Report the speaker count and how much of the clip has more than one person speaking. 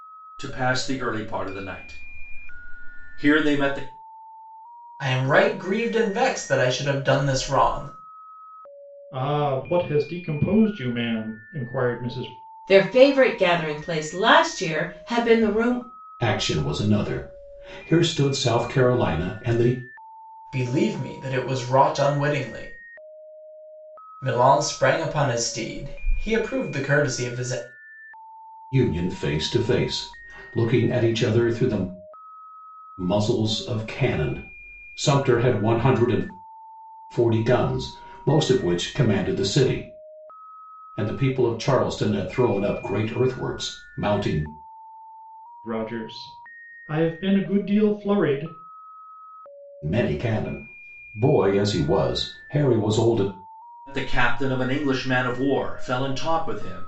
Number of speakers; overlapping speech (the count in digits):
5, no overlap